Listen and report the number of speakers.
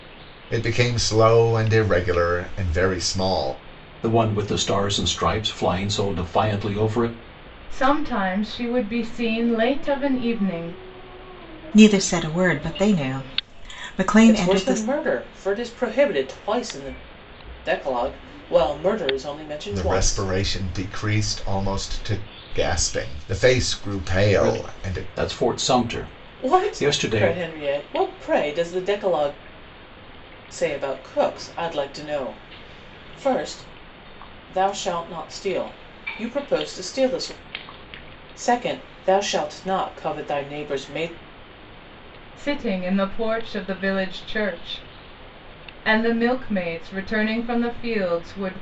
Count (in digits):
5